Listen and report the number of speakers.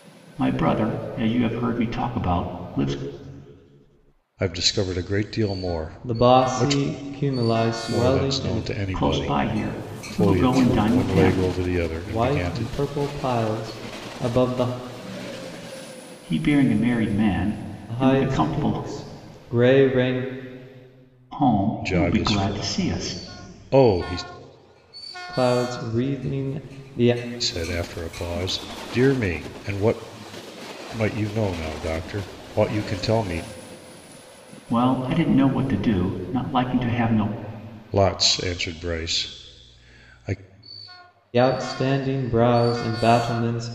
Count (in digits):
3